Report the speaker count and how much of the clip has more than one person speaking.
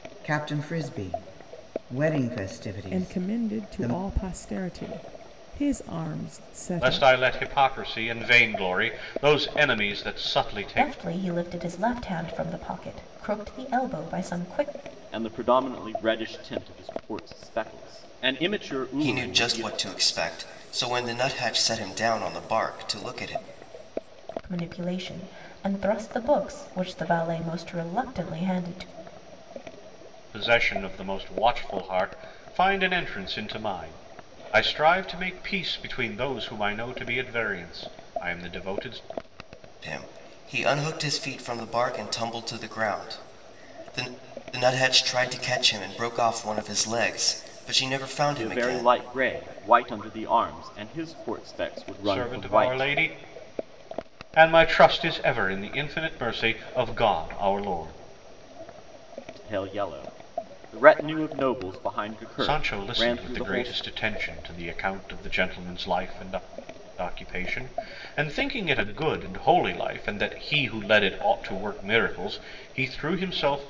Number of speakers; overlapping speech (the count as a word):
six, about 7%